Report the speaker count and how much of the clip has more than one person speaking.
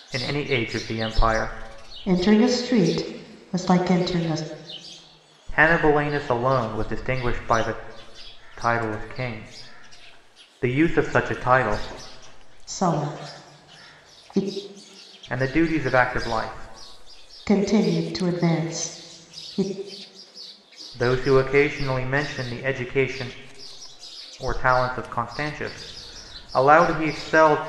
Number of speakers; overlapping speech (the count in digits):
2, no overlap